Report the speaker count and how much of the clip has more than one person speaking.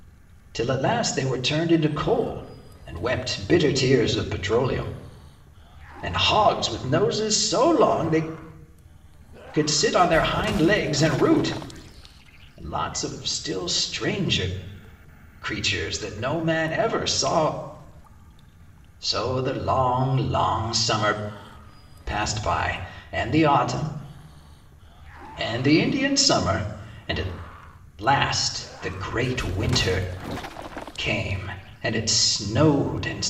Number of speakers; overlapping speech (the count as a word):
one, no overlap